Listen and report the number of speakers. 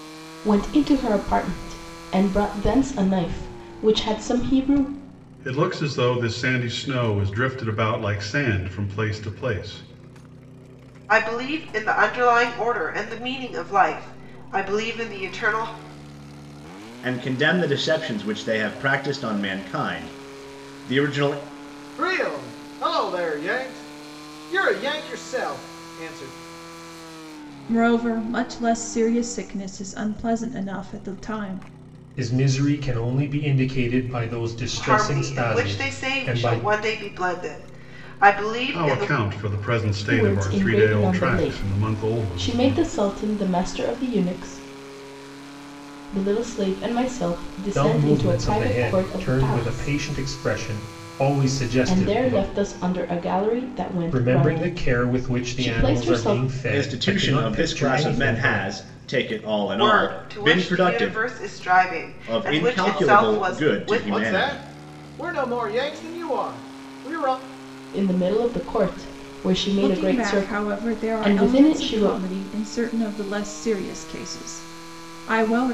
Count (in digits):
7